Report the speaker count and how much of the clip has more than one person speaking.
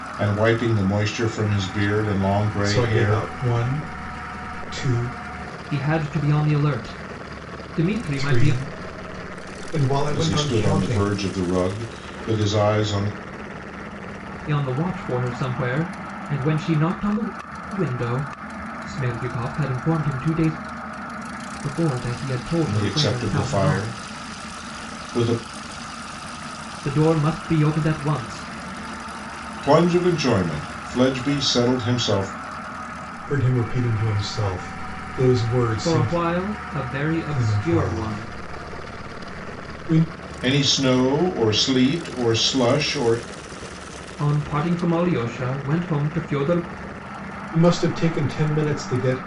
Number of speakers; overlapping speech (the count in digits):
3, about 10%